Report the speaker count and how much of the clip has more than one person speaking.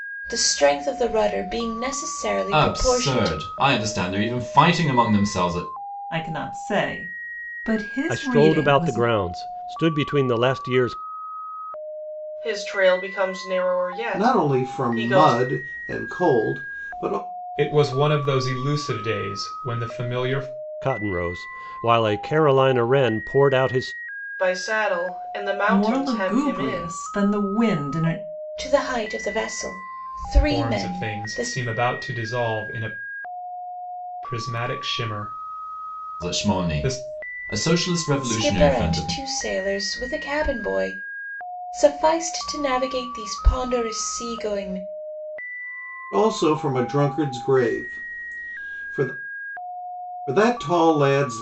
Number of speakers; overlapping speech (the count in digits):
7, about 14%